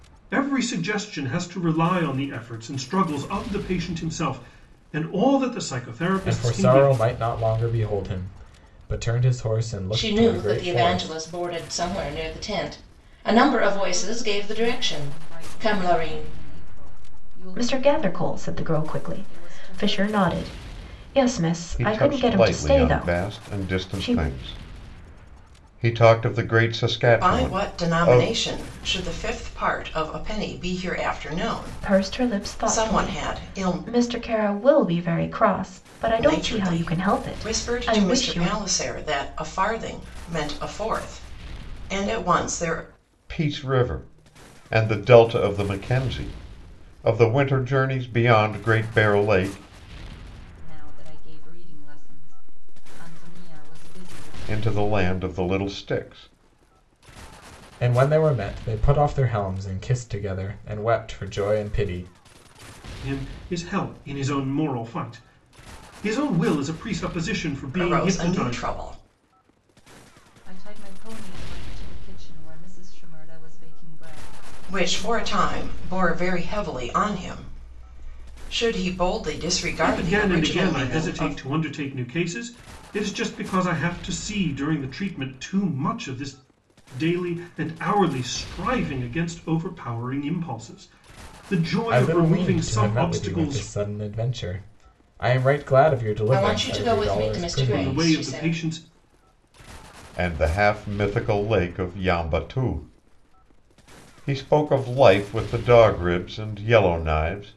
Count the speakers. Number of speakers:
7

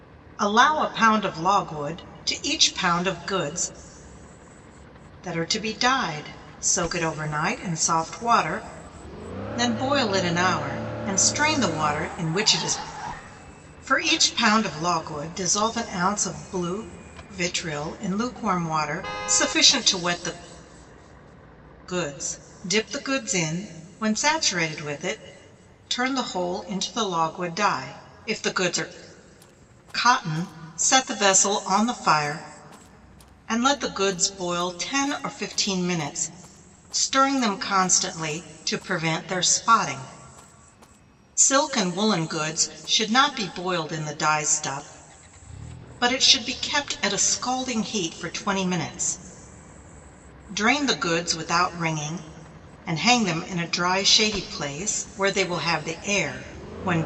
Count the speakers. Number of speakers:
1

